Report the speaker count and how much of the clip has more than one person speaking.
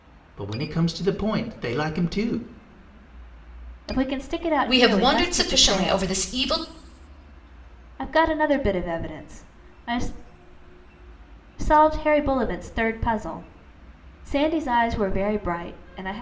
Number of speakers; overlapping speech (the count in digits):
3, about 9%